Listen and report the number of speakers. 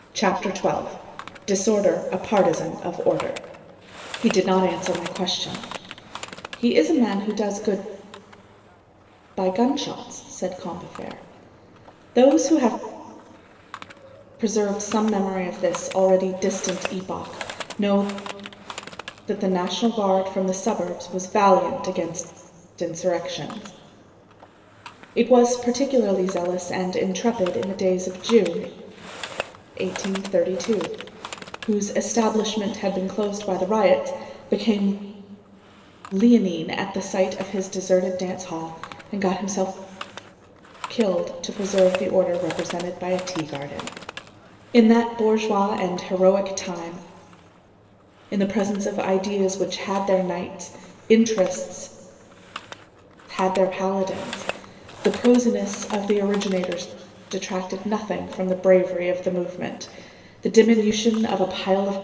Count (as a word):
one